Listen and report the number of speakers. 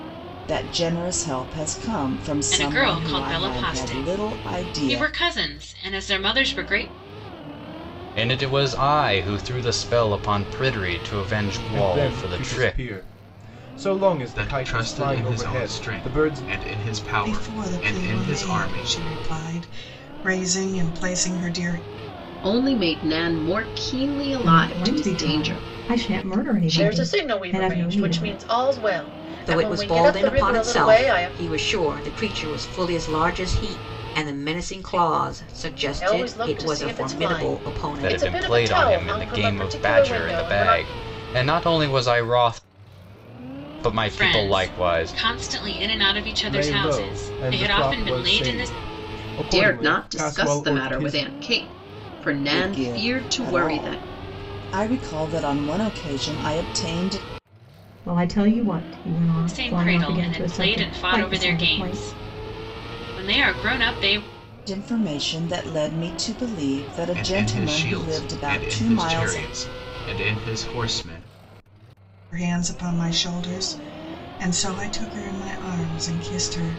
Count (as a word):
ten